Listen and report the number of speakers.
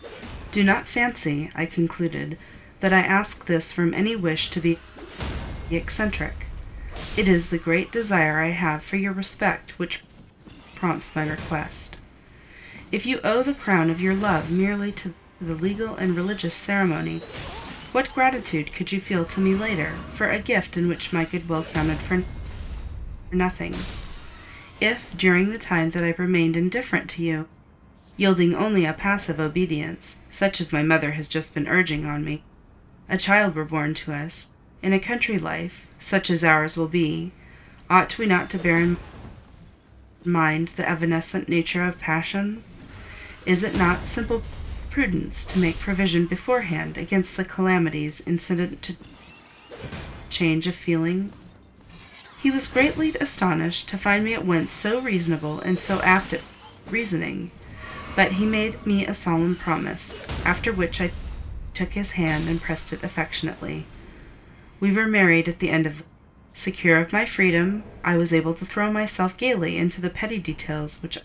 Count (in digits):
1